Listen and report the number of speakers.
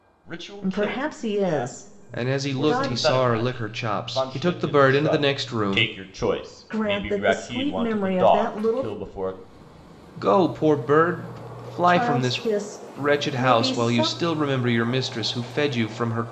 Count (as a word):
three